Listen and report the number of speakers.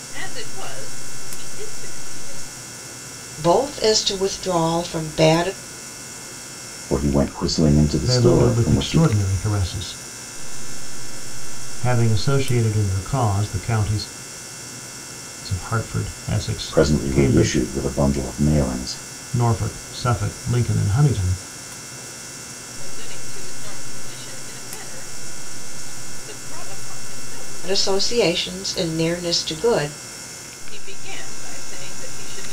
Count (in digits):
5